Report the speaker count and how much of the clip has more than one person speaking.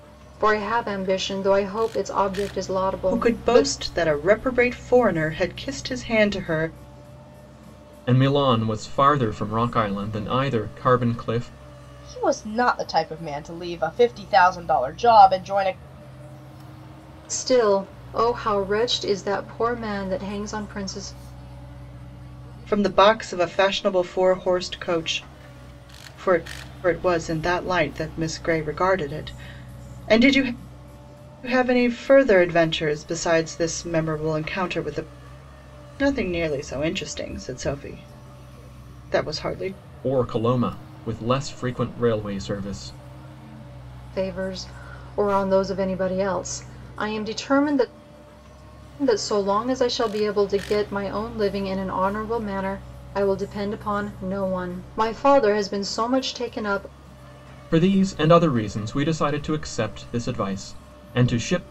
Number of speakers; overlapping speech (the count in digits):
4, about 1%